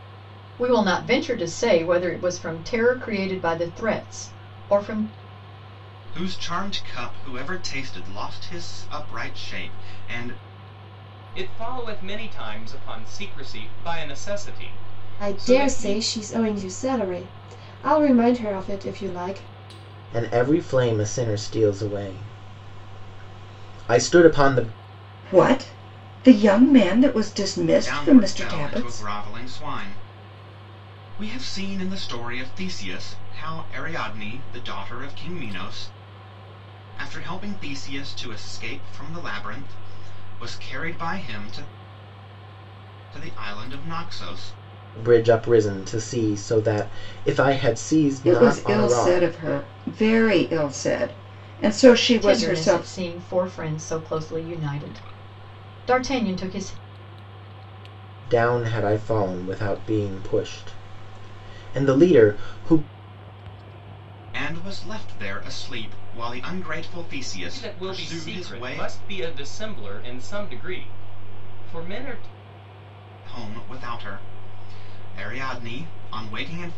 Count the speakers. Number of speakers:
6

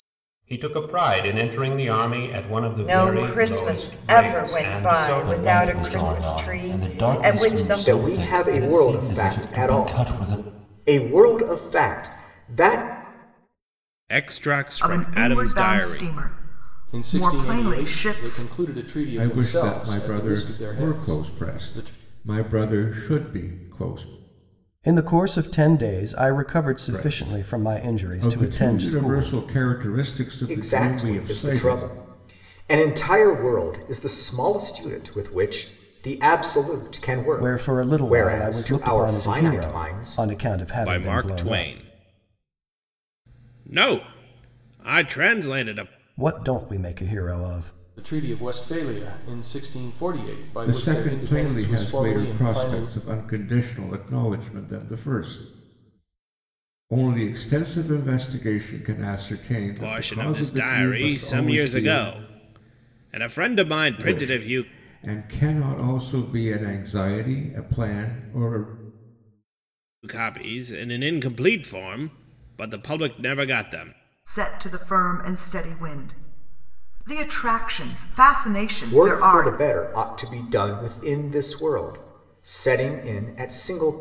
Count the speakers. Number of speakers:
9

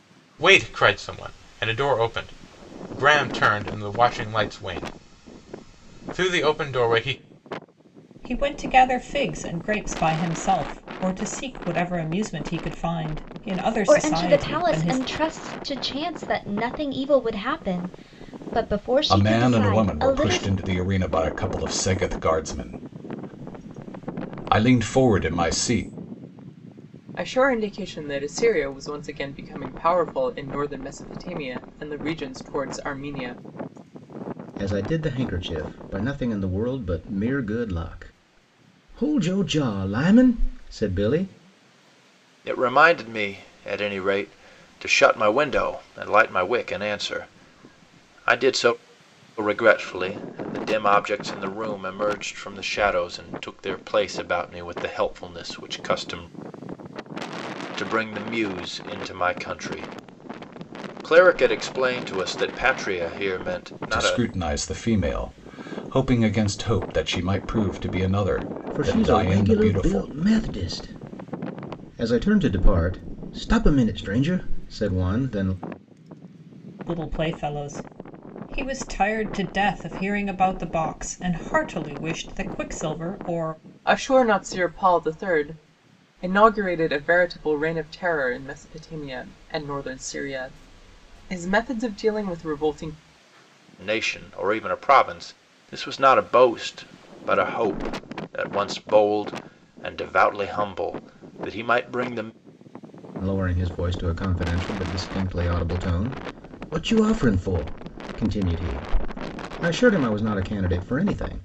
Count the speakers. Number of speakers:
7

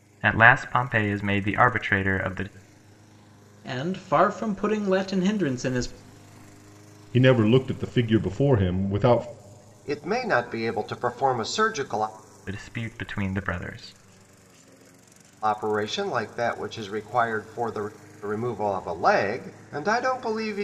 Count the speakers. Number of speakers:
4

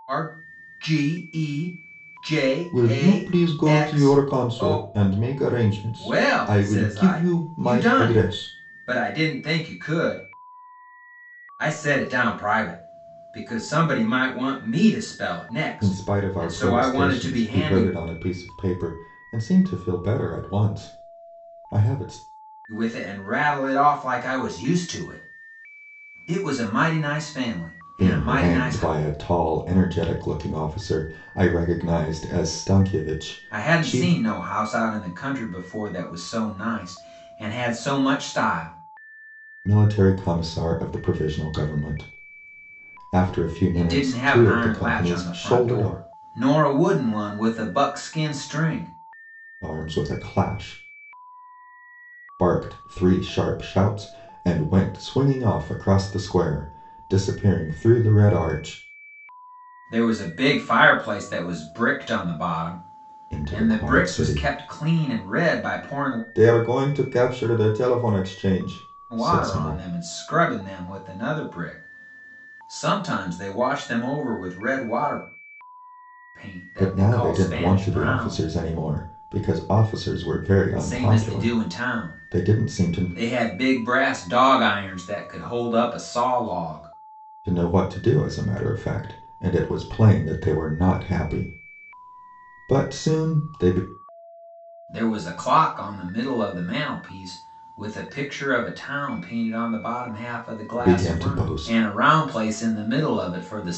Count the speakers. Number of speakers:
2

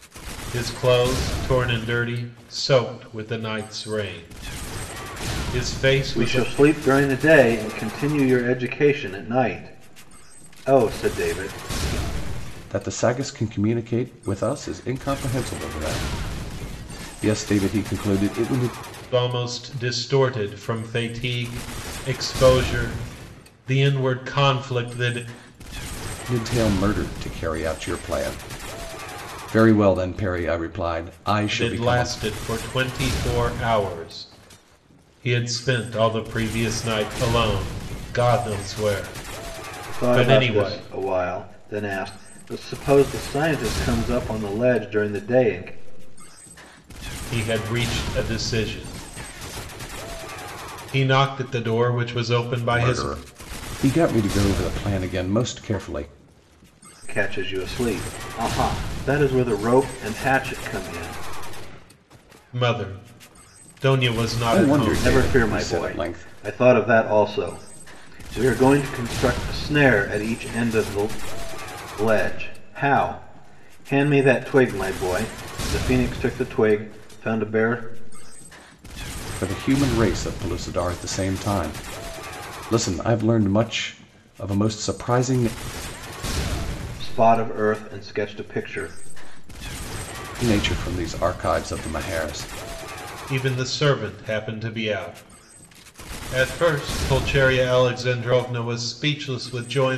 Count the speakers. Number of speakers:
3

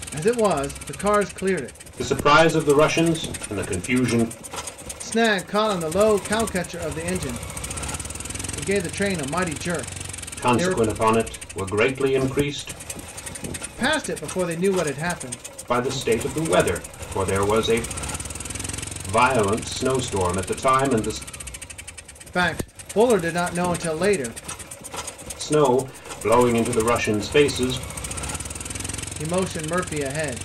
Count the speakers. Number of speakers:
2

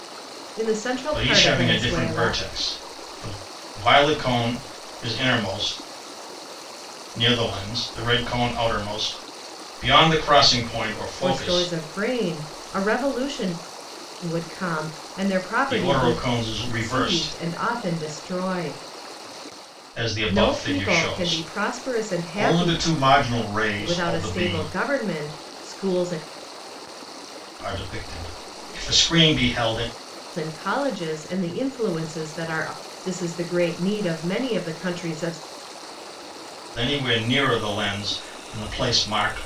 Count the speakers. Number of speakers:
2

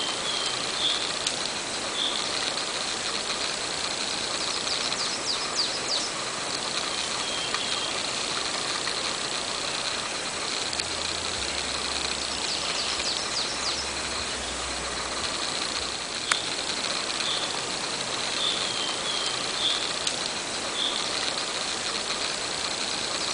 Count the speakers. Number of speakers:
0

